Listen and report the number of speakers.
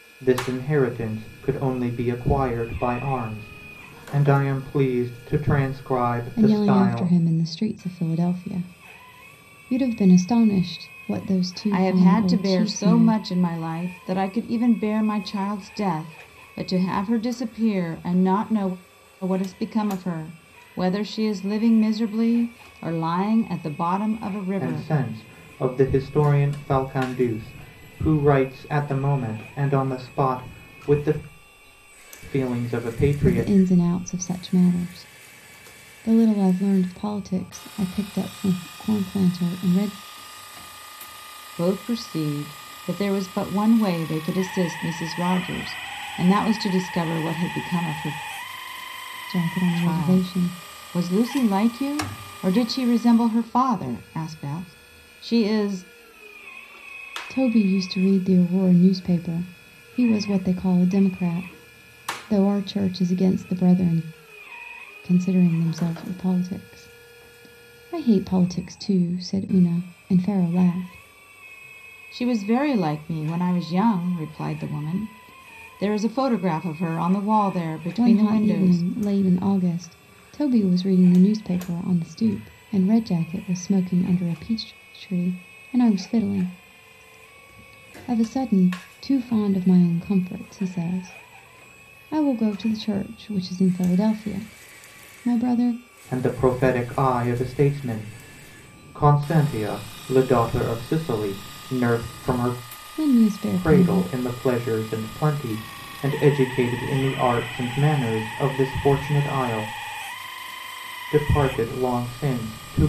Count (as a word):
three